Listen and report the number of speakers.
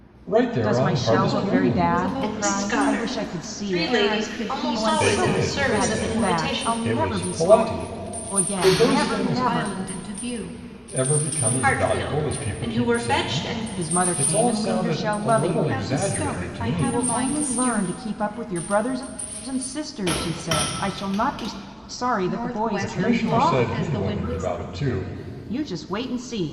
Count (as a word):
four